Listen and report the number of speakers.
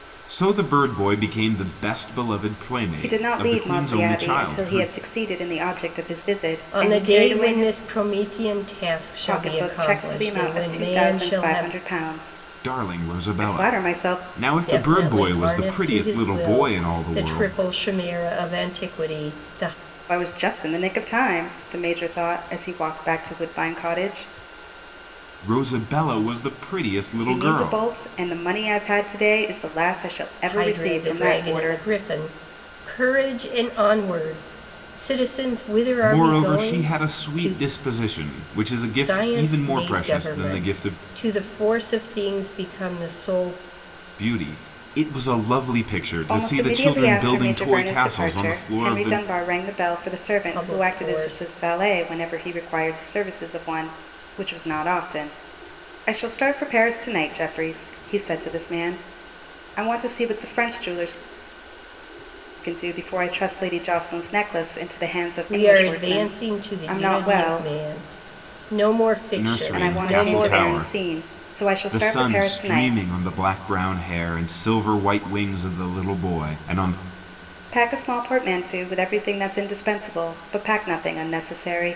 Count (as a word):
three